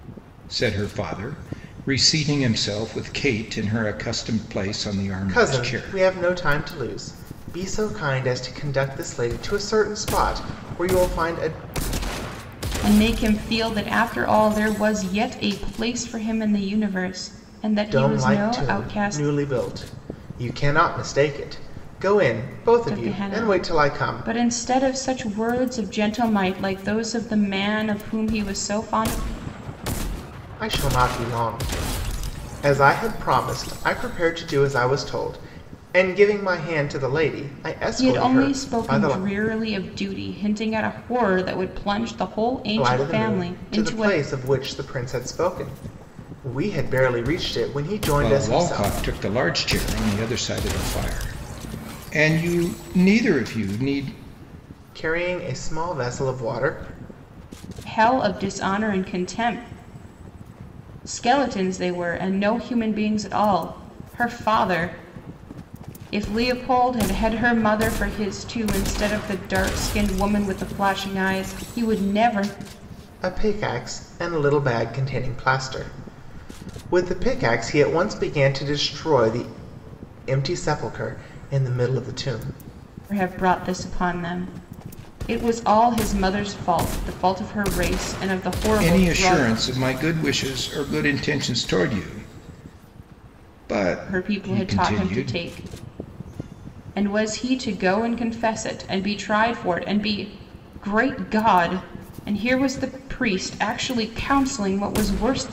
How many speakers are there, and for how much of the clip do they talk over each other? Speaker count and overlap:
3, about 9%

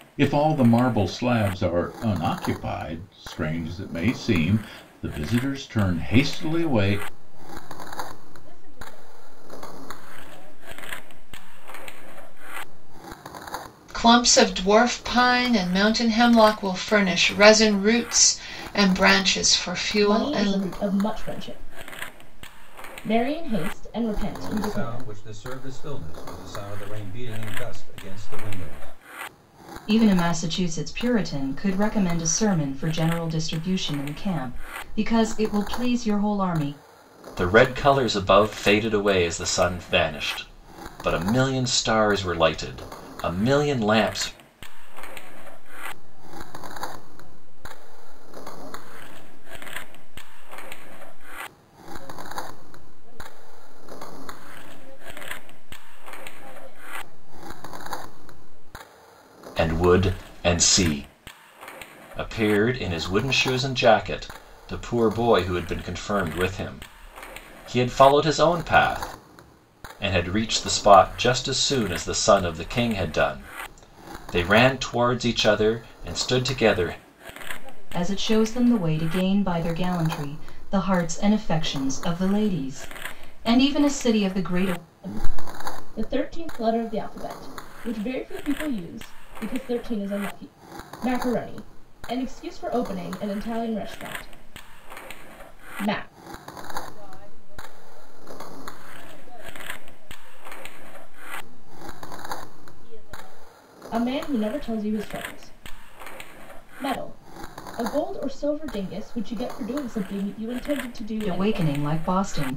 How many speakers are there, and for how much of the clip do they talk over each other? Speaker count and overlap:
7, about 3%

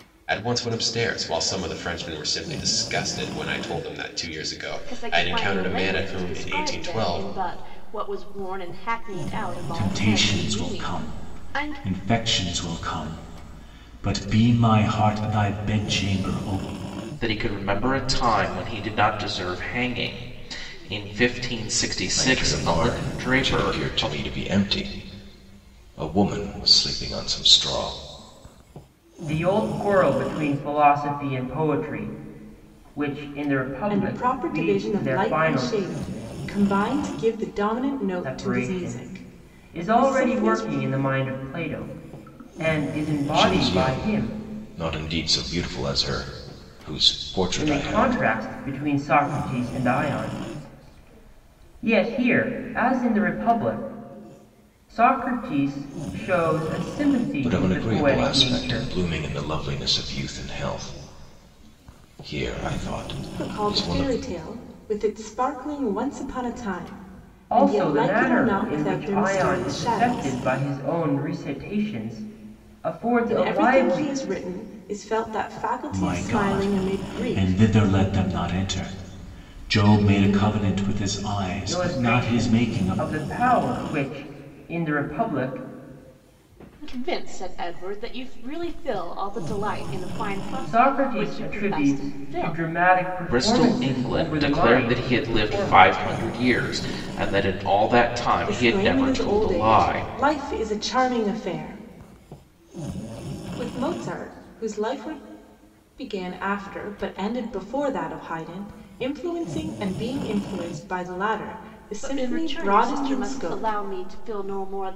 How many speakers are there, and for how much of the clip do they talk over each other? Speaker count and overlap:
7, about 27%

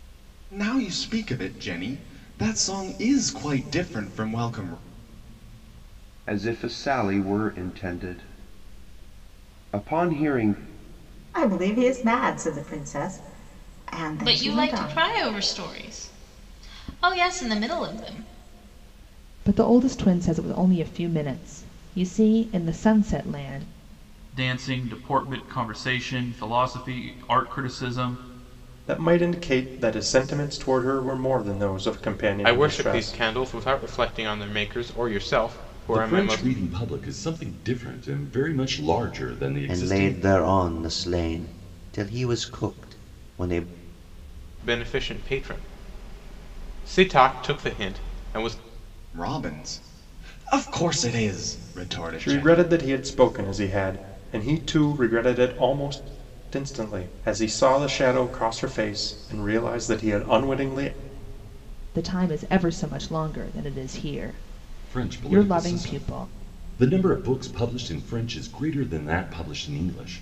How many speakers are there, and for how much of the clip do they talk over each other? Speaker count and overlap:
10, about 7%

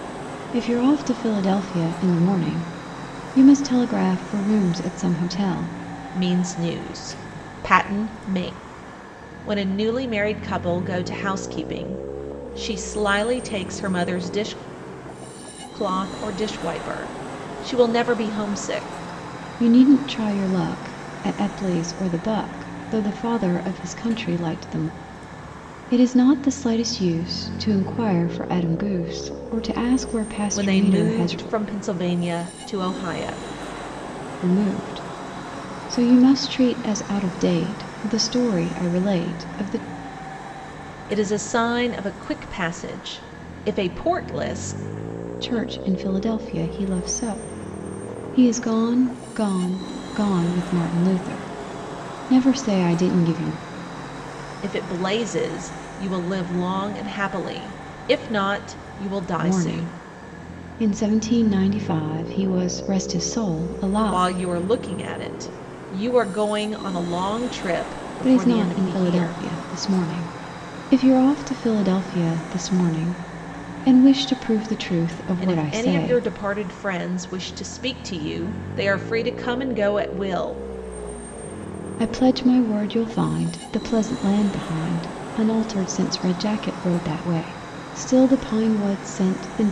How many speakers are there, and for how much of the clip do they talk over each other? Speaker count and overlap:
2, about 5%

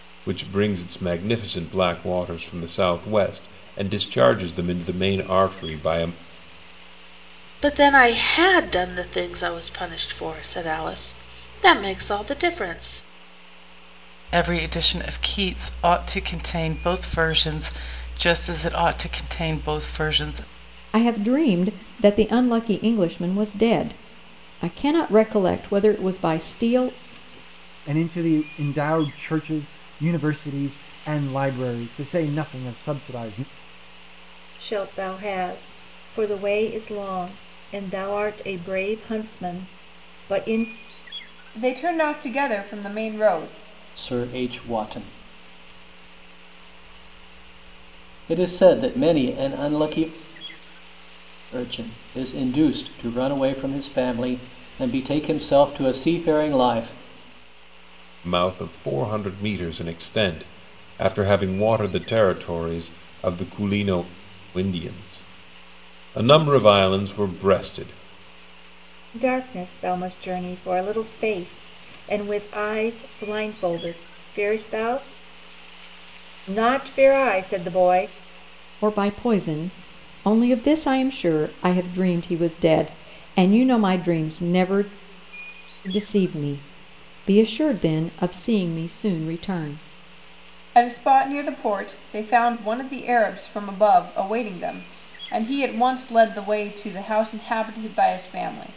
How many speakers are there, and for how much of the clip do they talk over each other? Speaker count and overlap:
8, no overlap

